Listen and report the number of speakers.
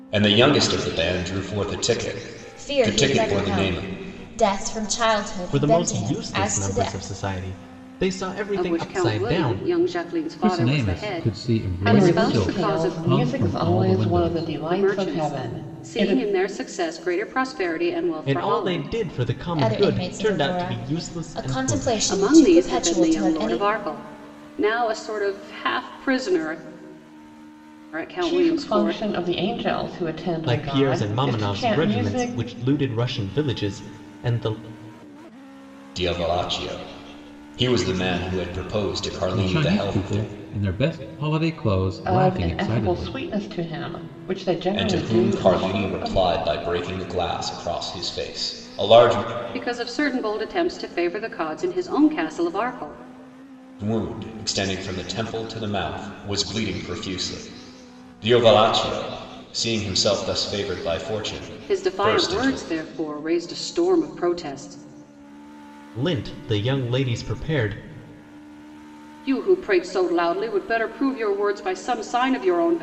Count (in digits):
6